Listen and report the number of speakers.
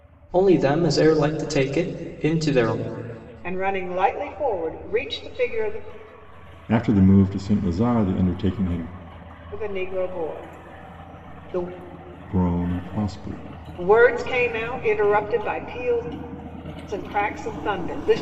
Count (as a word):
three